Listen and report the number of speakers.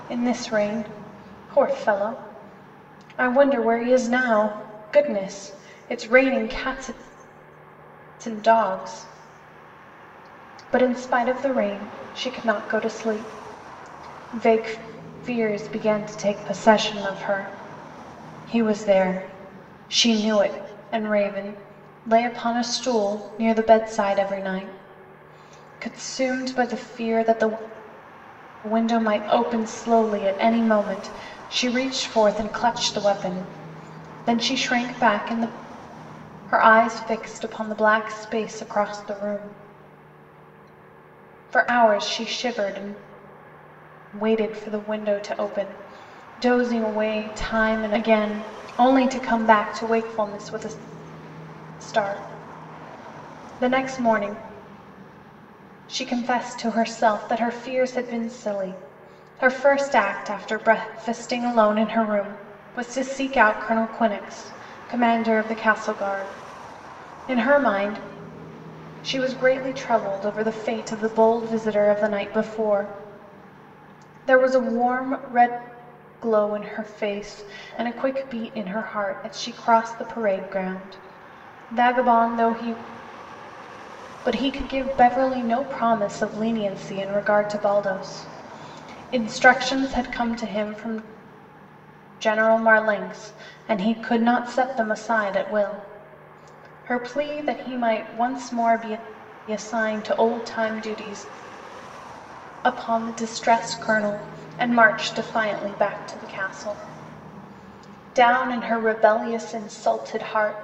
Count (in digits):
1